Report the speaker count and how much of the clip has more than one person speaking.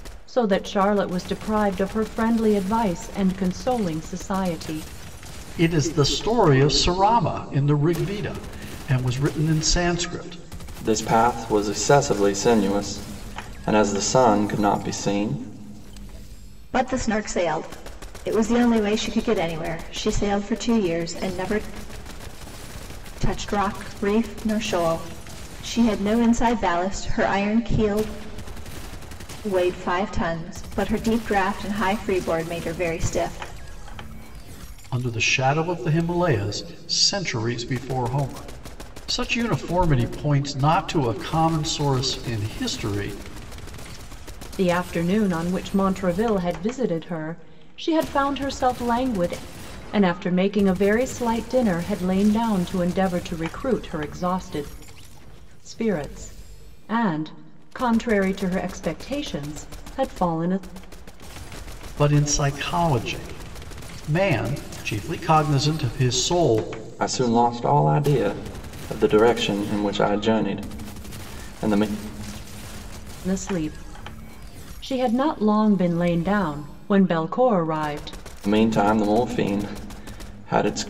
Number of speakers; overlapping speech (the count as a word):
four, no overlap